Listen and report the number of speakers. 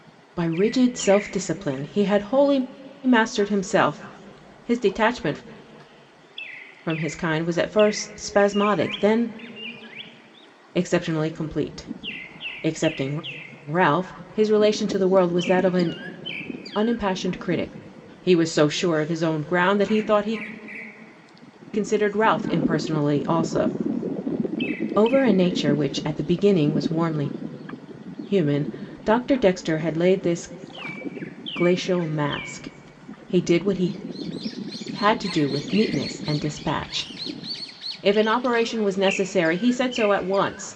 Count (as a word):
one